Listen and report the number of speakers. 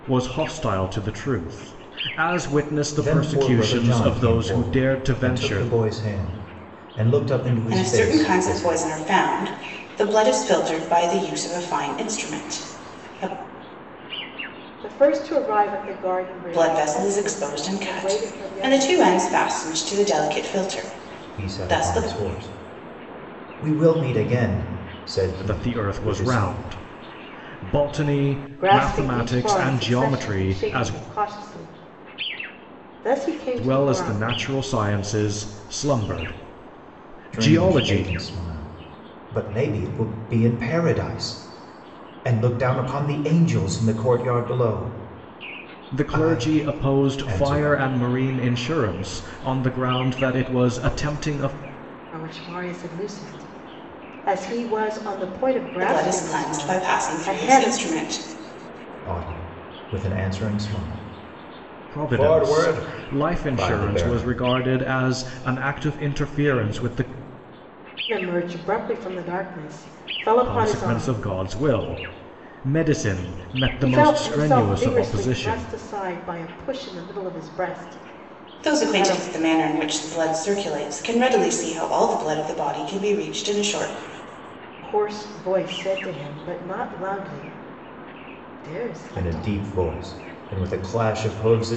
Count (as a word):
four